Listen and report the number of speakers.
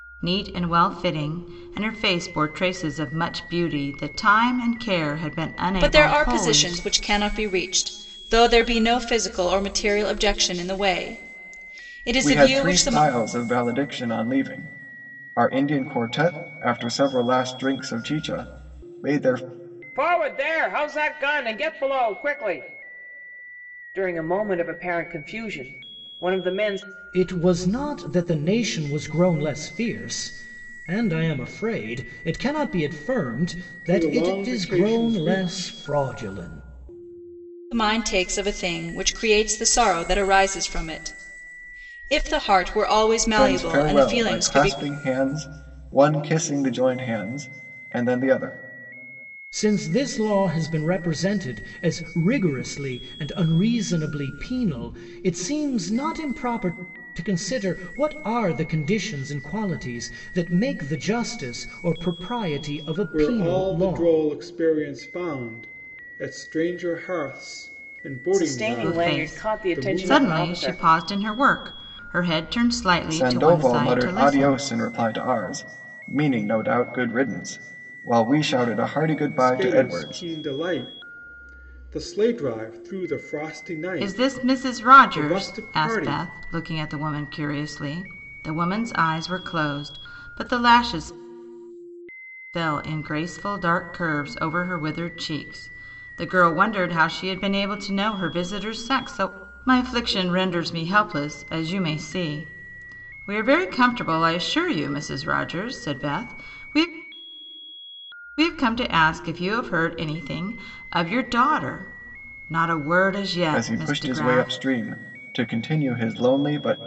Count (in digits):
6